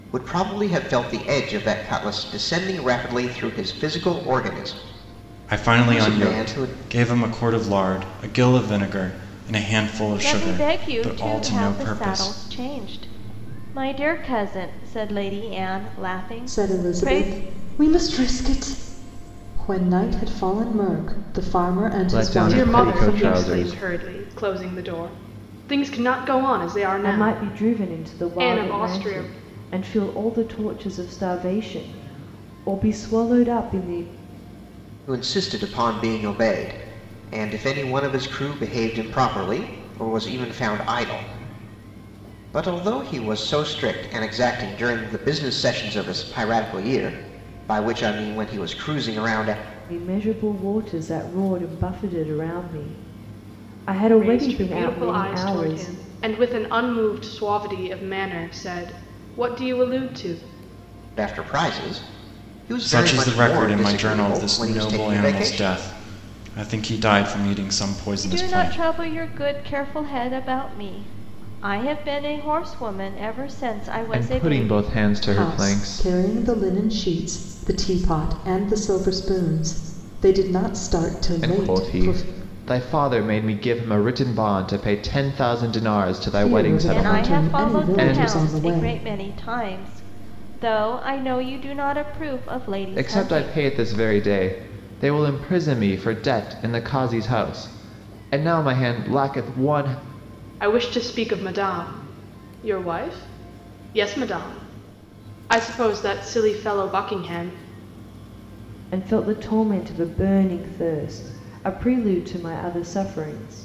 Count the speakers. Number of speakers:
seven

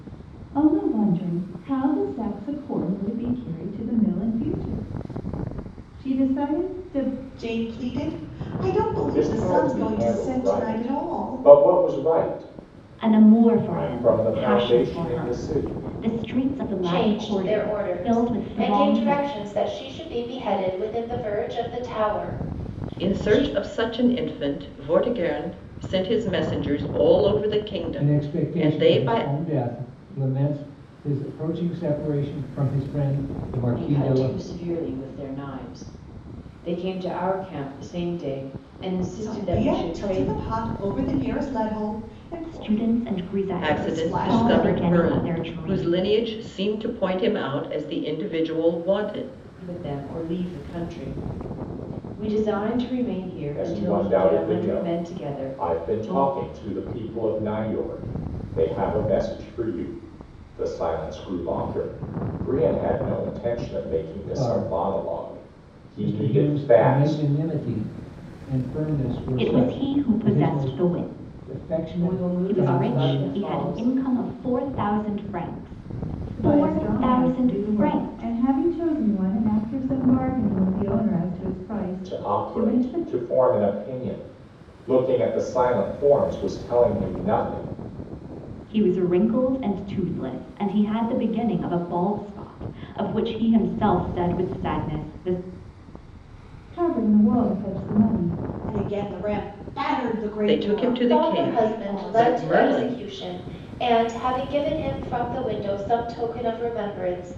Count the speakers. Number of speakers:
eight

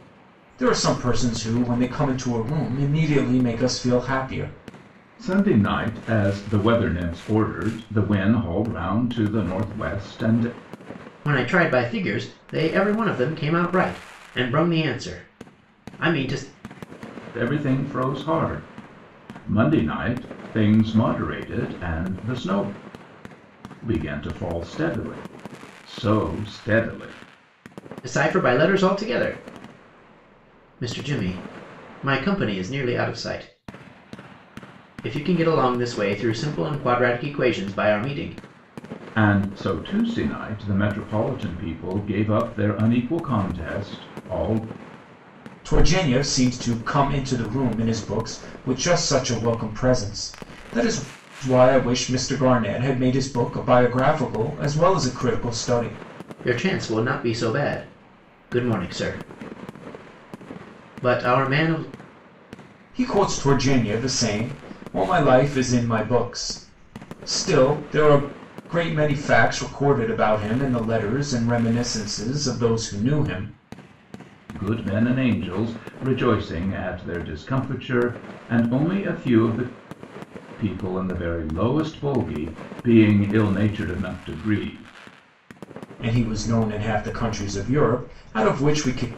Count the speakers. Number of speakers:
three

